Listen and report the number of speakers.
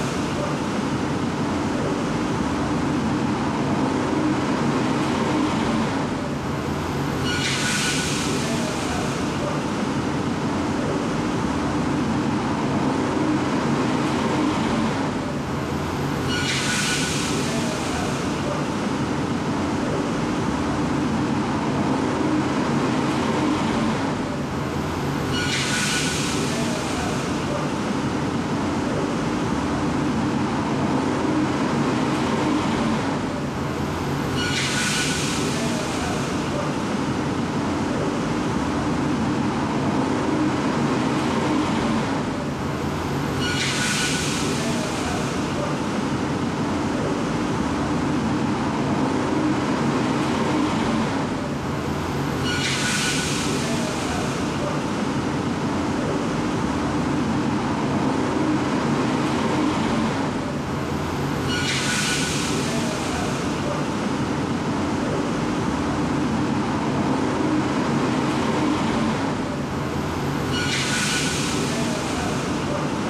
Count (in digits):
0